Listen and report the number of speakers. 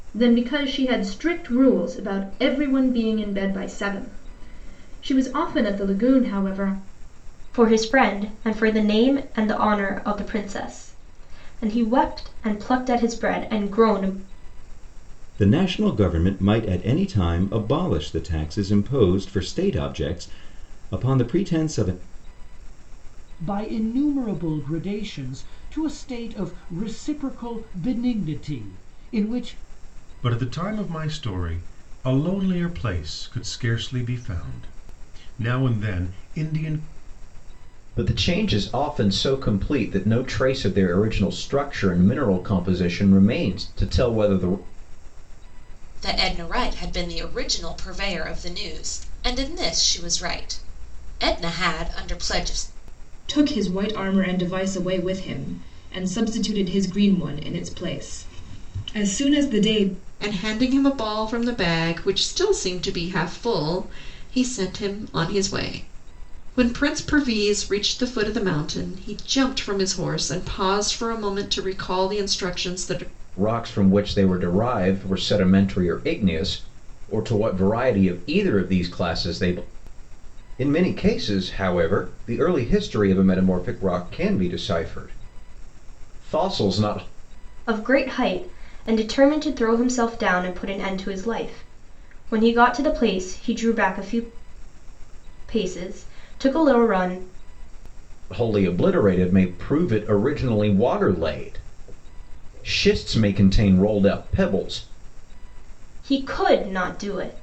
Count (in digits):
9